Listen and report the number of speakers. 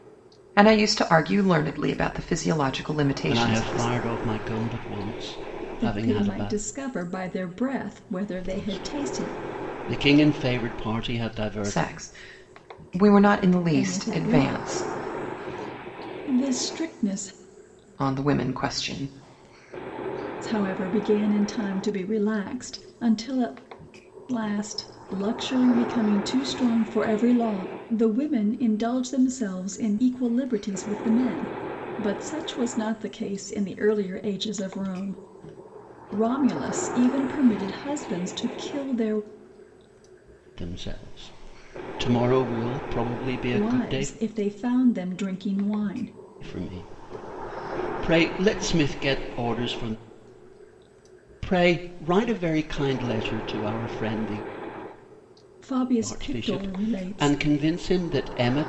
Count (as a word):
three